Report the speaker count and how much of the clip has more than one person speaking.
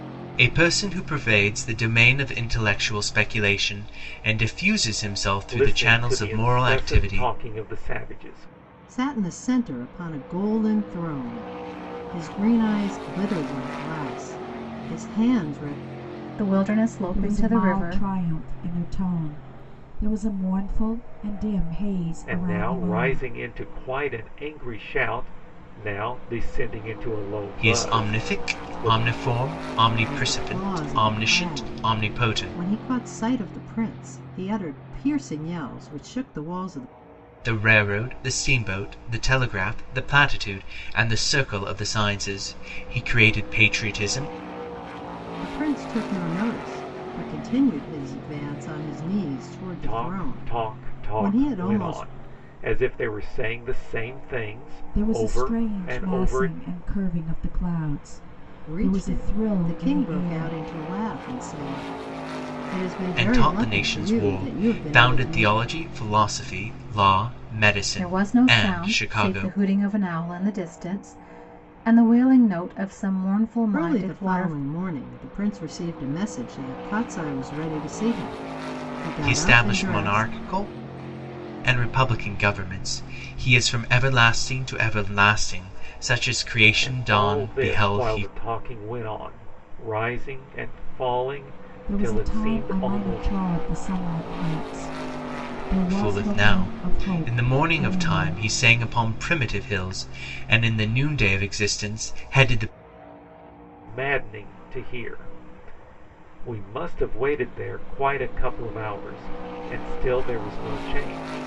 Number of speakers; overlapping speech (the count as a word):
five, about 23%